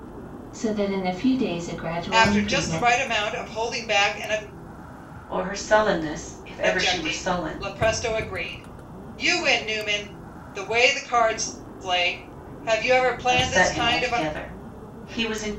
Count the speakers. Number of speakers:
three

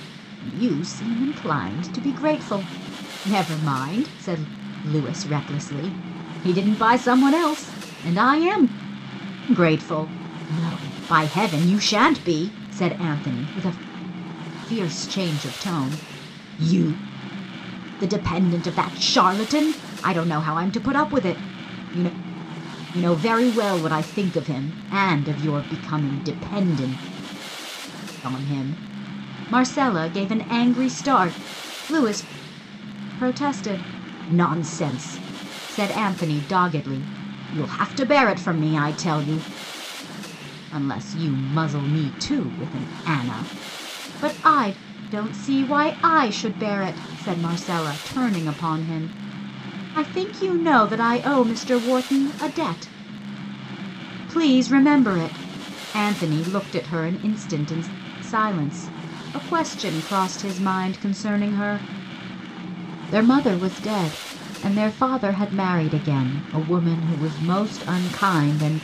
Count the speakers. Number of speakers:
one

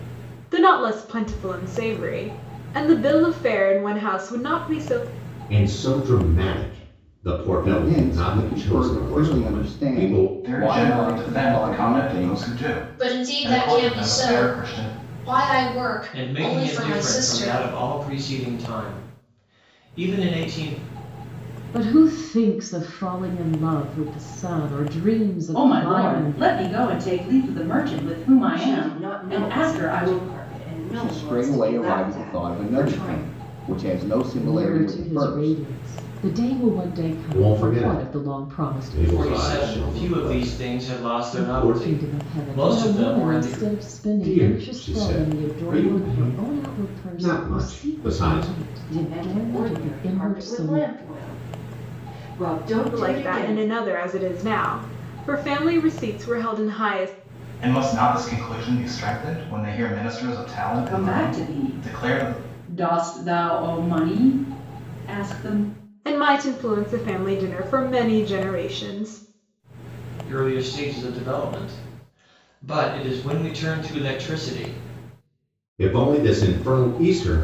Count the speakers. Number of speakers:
nine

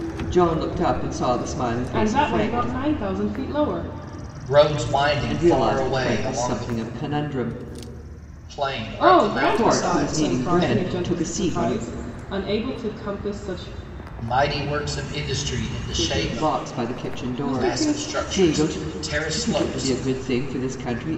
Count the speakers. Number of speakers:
three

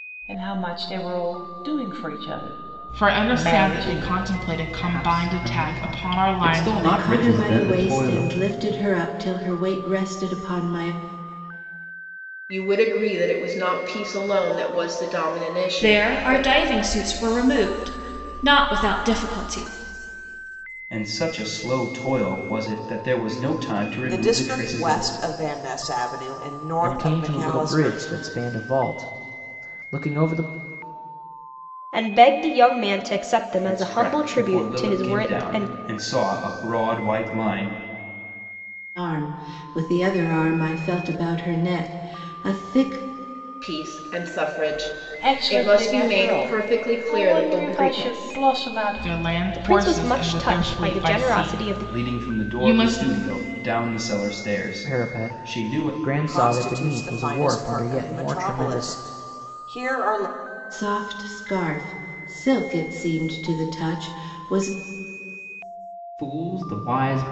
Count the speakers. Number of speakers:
ten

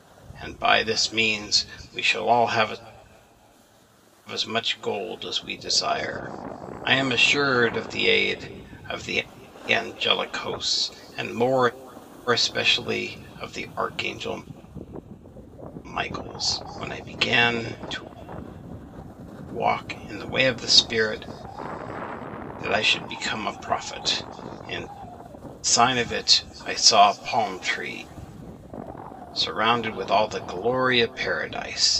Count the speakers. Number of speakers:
one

